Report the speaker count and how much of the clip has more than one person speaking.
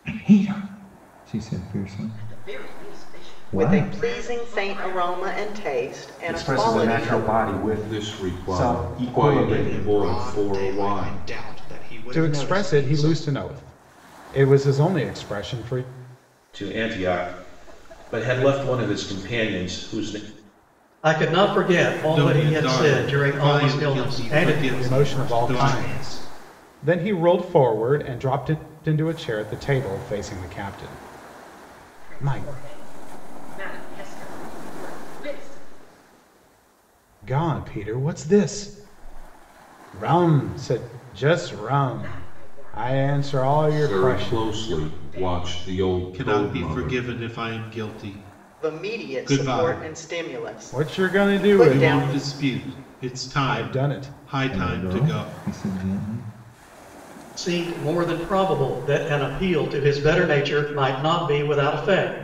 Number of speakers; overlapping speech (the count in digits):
10, about 39%